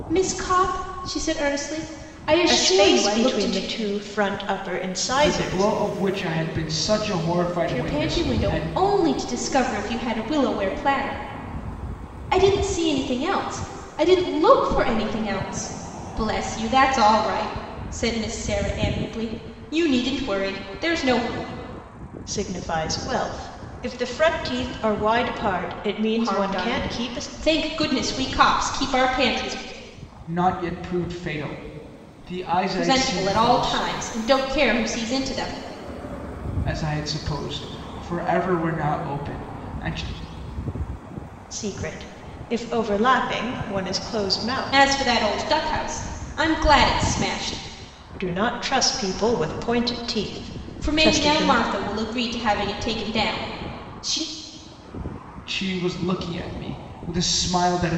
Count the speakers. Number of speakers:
3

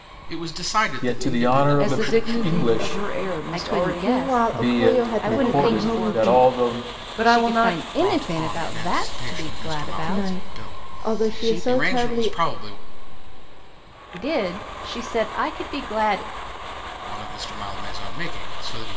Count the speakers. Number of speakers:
5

